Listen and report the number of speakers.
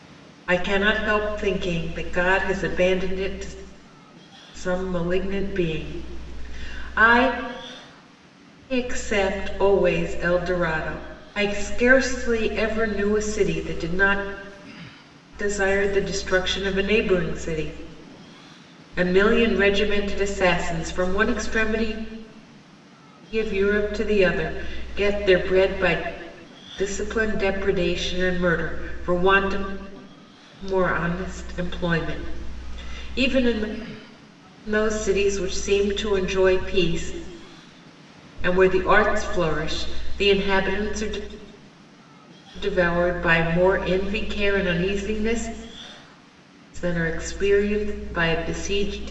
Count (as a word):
one